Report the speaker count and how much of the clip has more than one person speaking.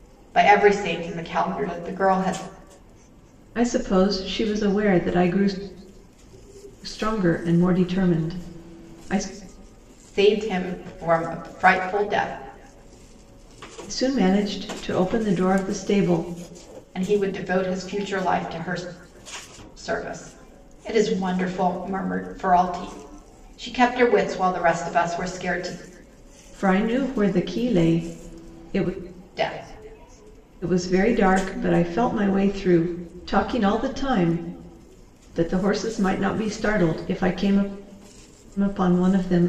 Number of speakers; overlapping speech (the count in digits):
2, no overlap